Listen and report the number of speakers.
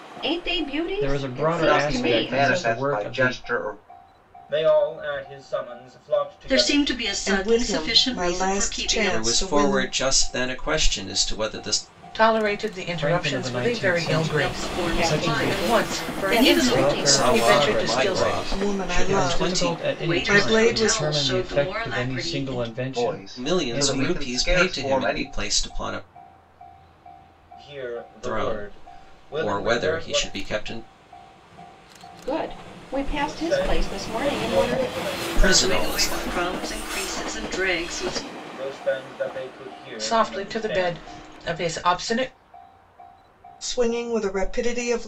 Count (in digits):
8